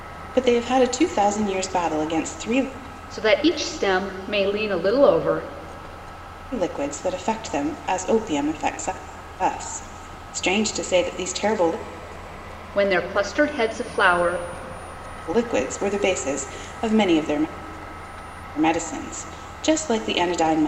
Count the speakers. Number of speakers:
2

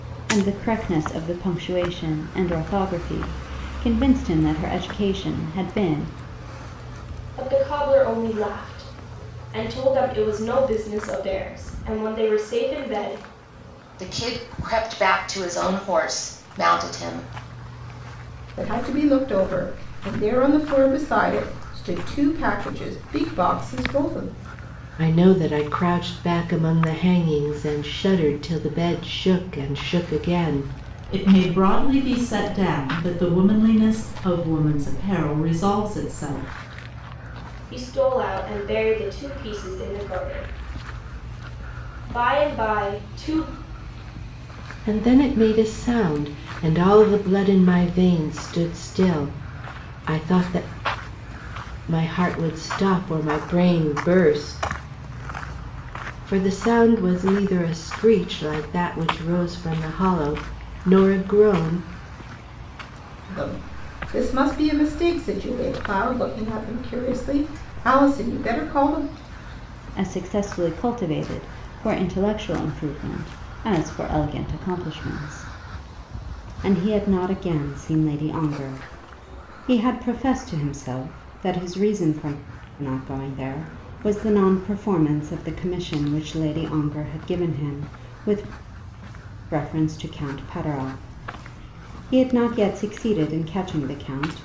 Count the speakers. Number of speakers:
6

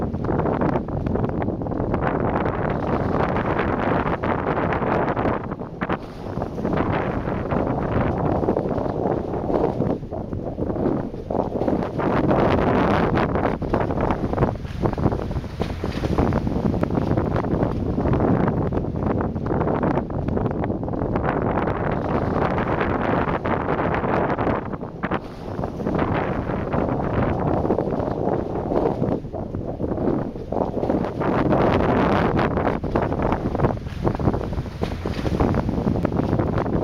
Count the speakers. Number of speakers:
0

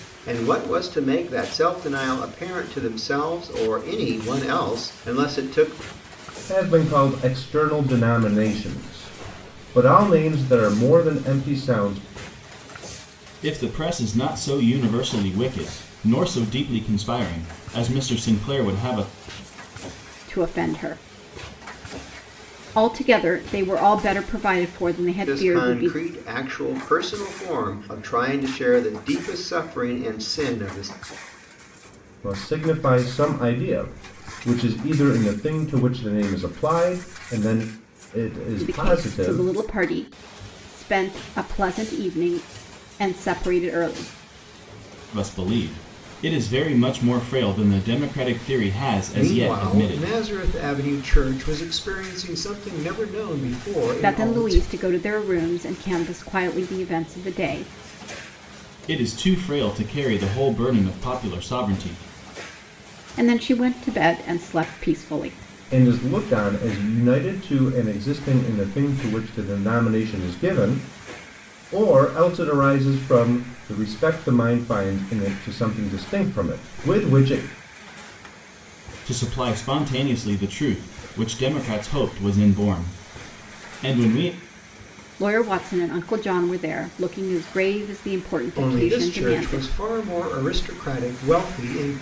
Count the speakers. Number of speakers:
4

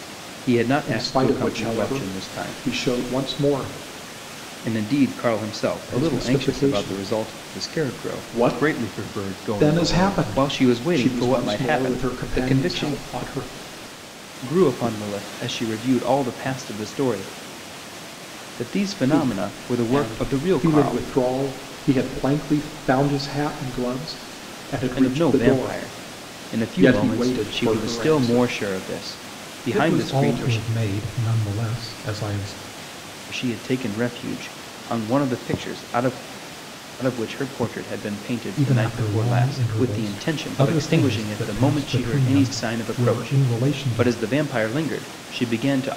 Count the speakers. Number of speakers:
2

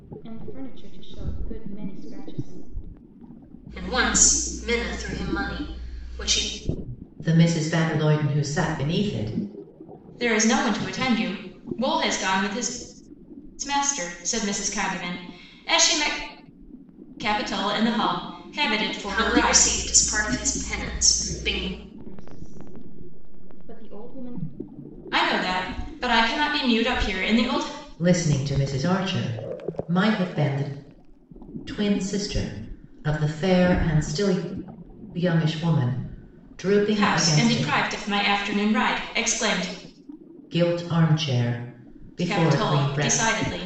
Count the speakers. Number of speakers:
4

